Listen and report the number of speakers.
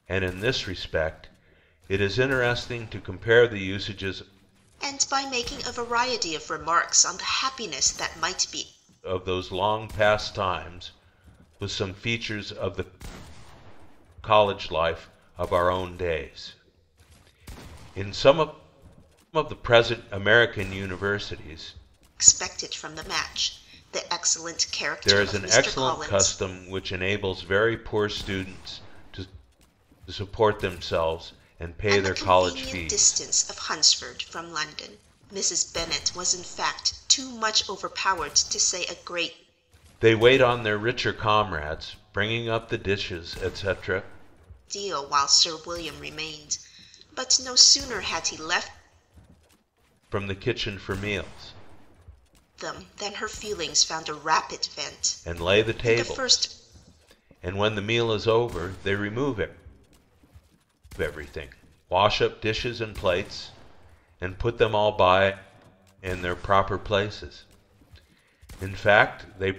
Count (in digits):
2